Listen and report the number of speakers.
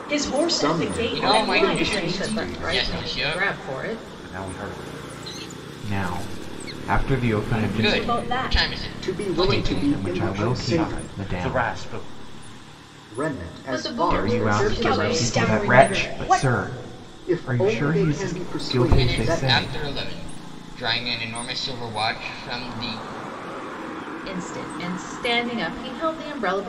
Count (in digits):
6